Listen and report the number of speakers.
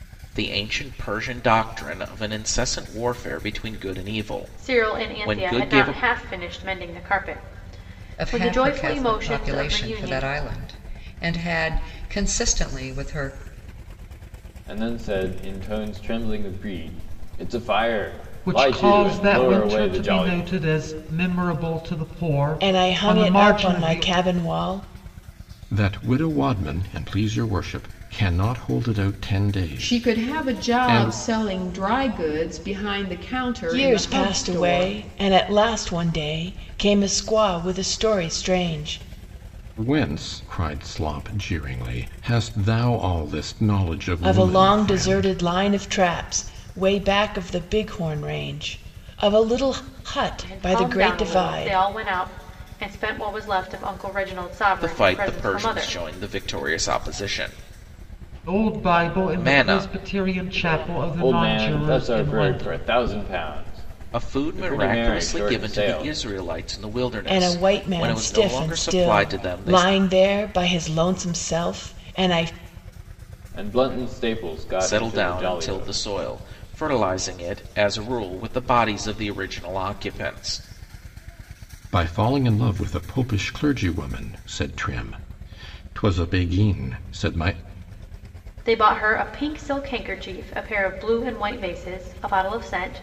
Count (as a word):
eight